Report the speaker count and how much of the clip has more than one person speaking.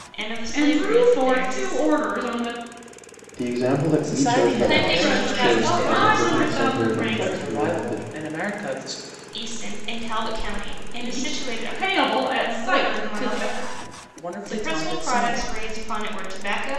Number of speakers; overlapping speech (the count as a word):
four, about 51%